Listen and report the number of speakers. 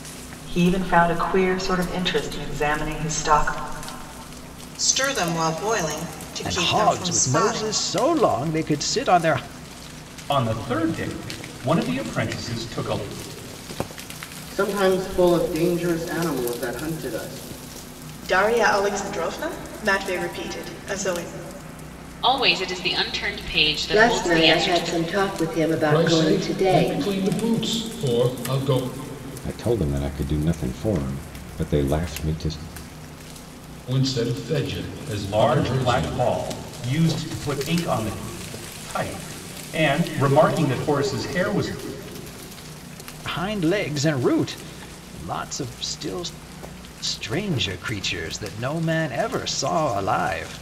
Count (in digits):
10